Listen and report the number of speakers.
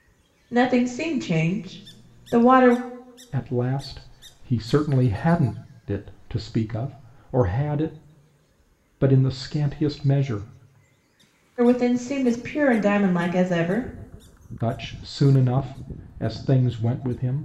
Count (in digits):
2